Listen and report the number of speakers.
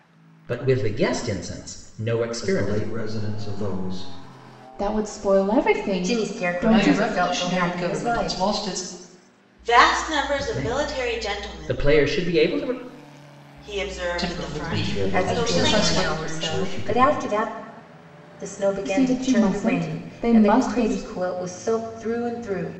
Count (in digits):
6